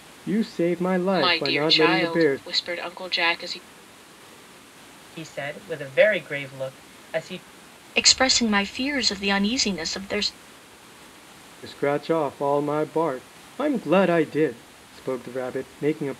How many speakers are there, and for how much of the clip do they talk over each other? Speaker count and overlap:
four, about 8%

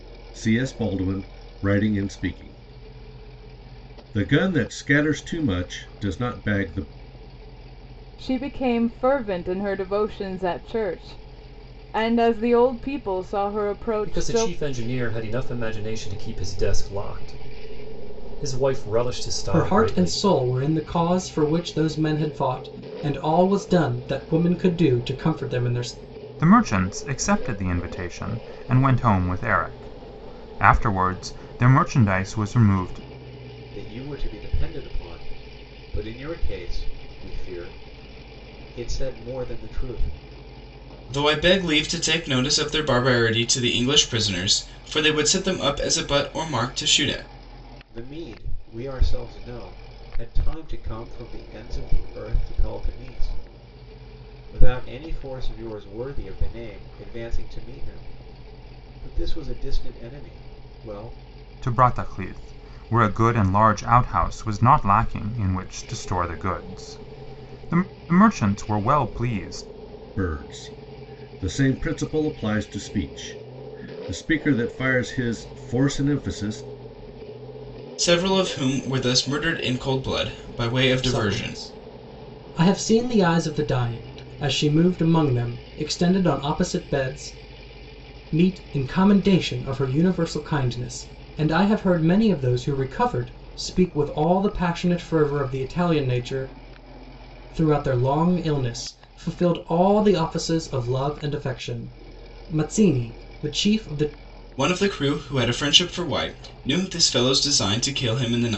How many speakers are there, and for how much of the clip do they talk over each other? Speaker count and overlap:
seven, about 2%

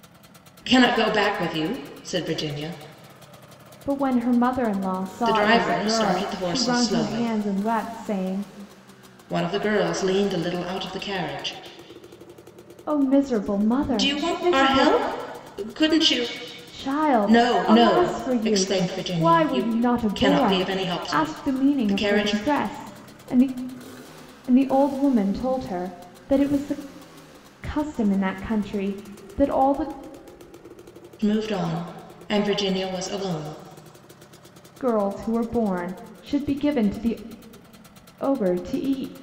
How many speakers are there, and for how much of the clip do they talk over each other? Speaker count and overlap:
two, about 18%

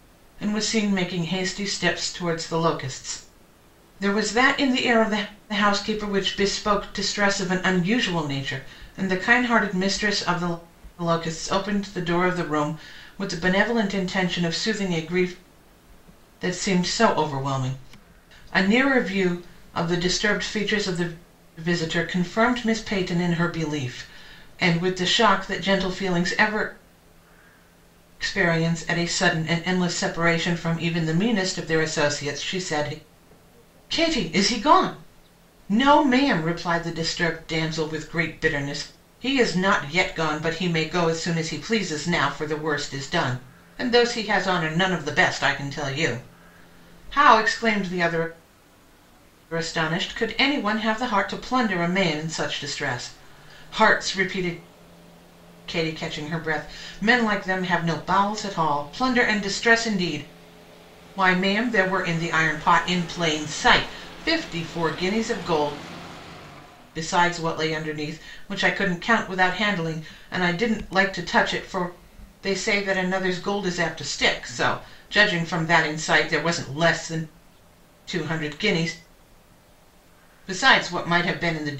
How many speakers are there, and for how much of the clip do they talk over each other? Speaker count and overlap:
one, no overlap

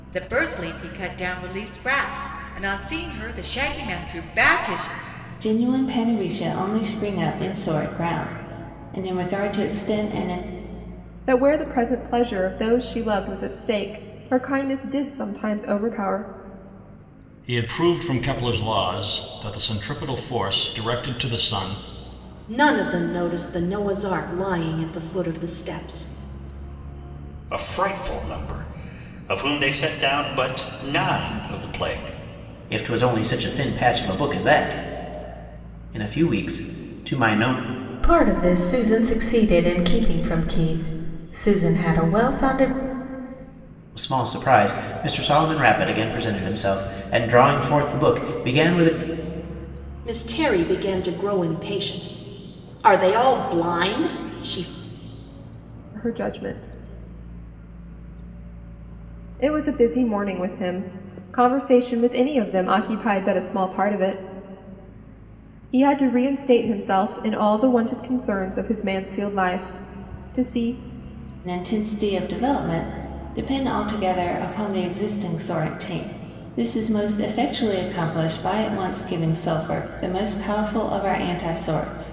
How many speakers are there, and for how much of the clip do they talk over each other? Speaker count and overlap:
eight, no overlap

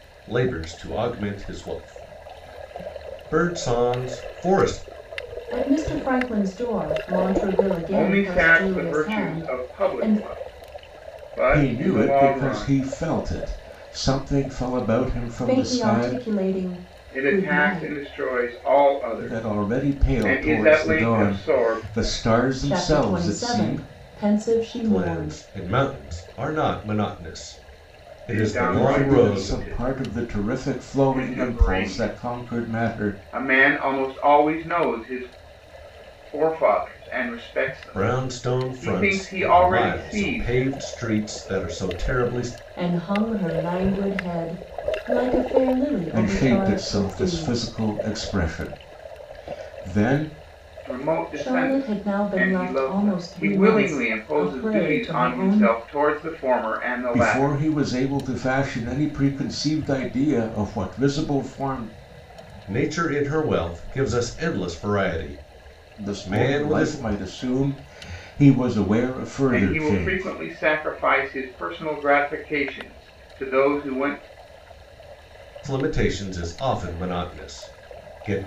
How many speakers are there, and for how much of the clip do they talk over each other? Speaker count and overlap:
four, about 32%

